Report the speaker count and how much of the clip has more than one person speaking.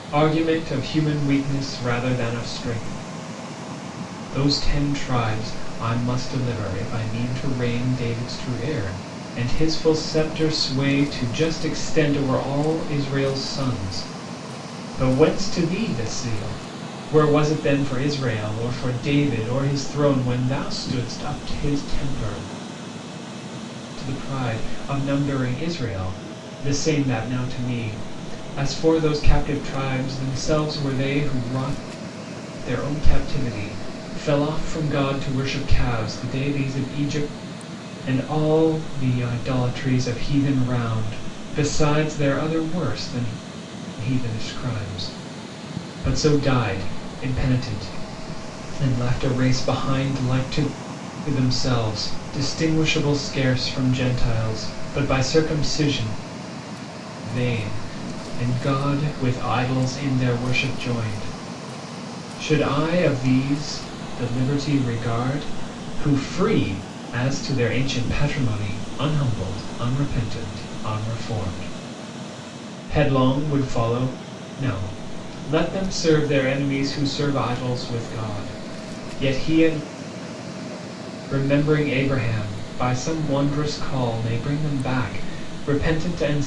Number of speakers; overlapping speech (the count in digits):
1, no overlap